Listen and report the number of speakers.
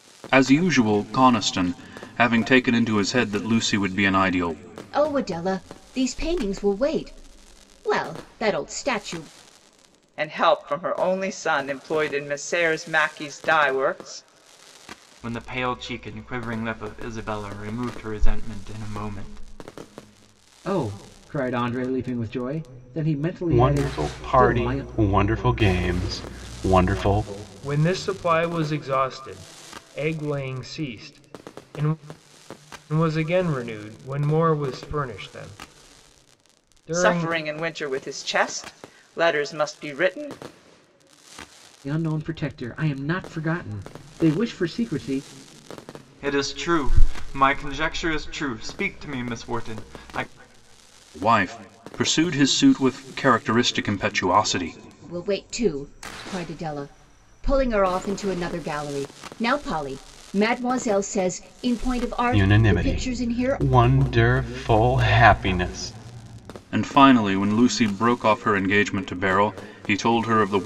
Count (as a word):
seven